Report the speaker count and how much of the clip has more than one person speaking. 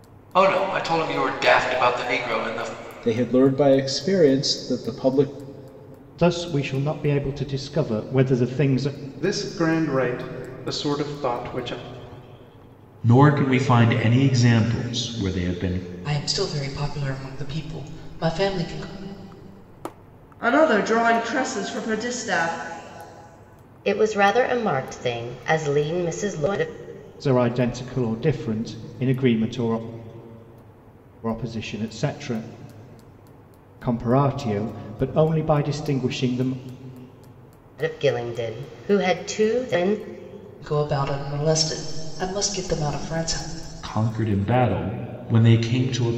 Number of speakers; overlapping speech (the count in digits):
8, no overlap